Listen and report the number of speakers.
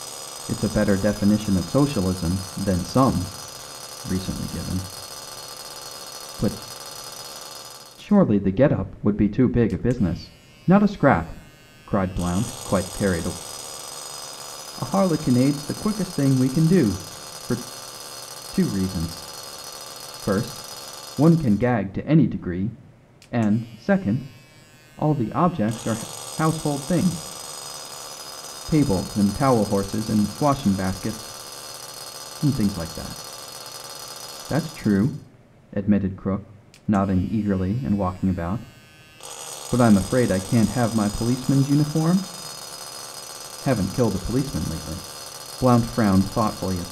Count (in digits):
1